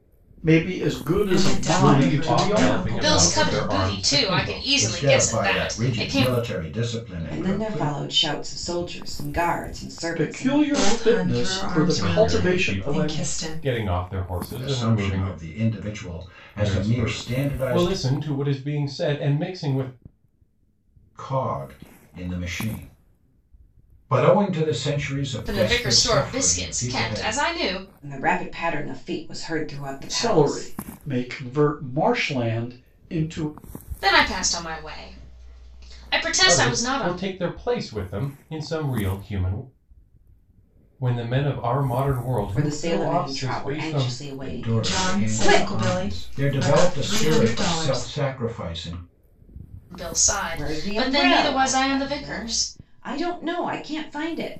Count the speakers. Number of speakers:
six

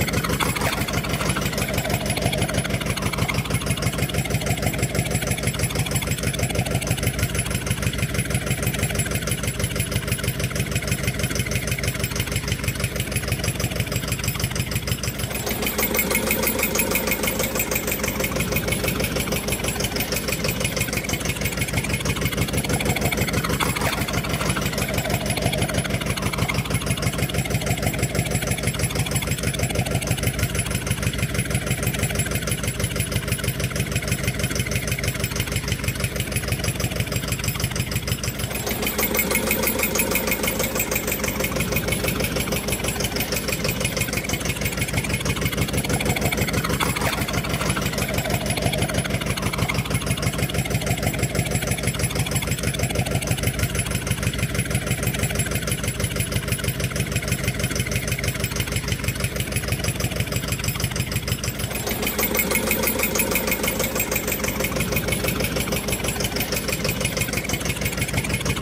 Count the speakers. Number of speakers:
zero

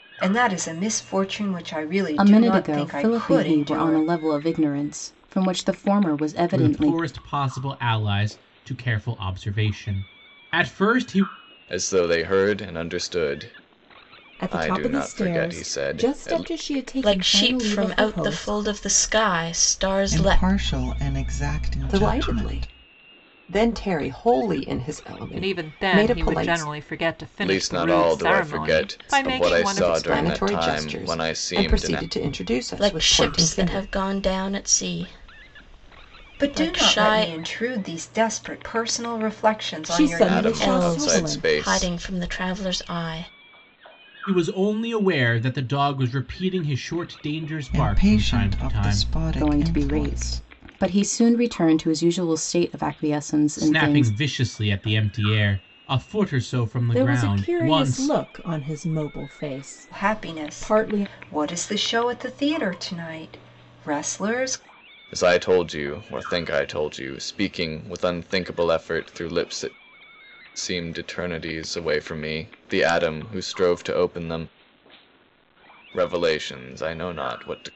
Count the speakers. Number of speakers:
nine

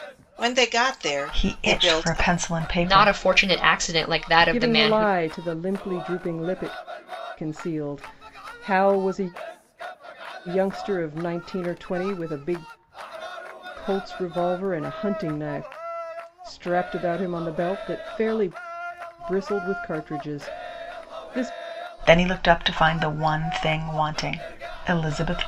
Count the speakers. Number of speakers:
four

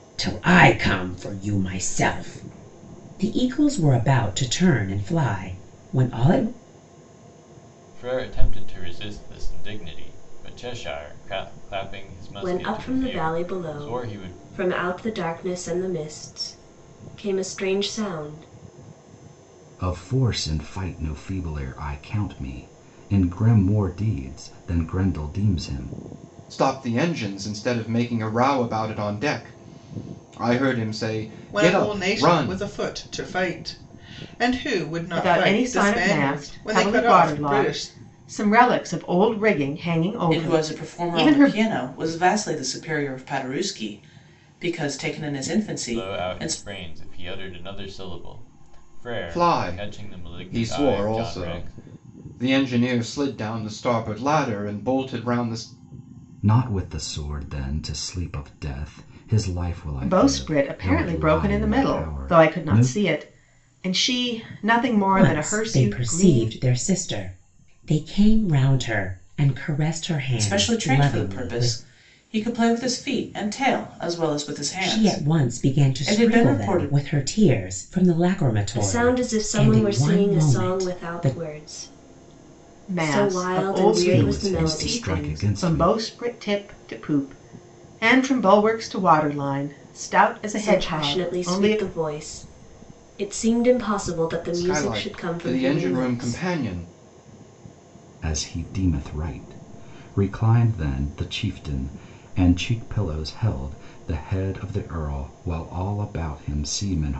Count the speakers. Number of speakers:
eight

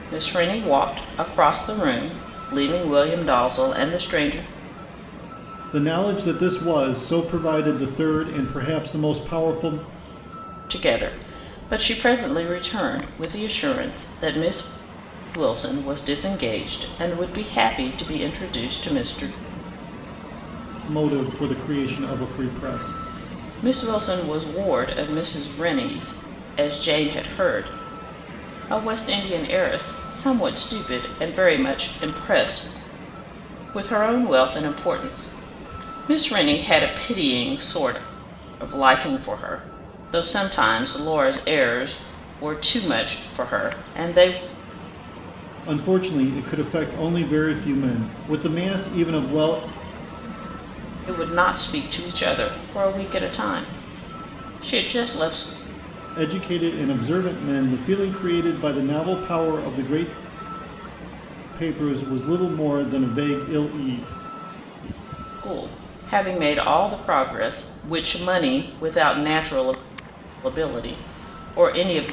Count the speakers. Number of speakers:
two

